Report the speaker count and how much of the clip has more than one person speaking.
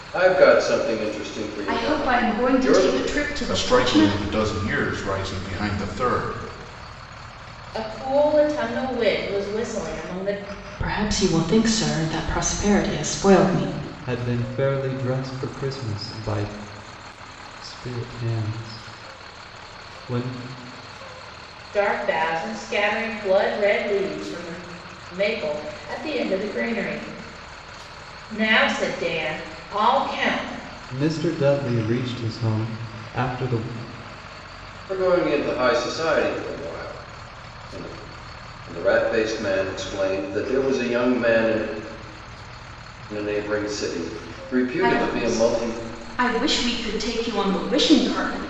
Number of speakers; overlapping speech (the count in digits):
6, about 6%